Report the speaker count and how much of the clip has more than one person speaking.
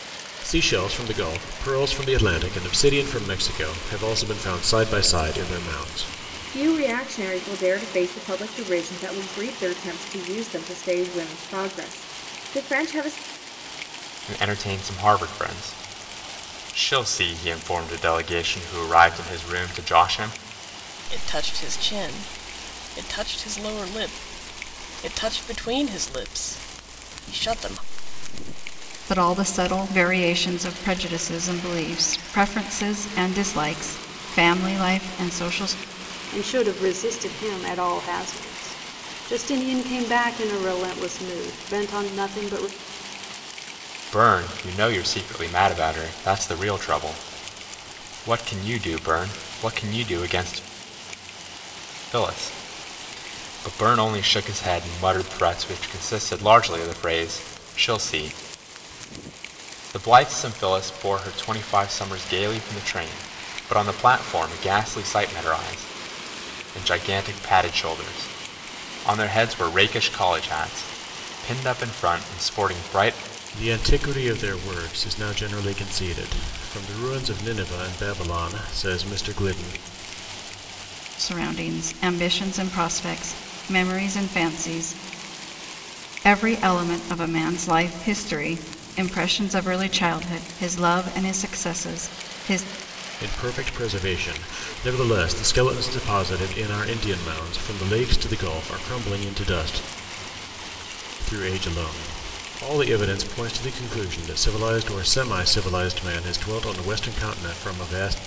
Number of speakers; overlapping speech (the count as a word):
six, no overlap